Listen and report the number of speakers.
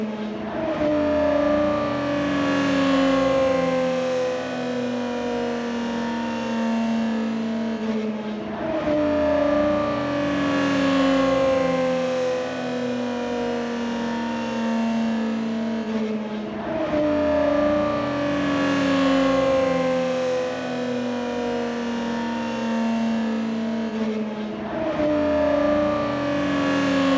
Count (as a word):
zero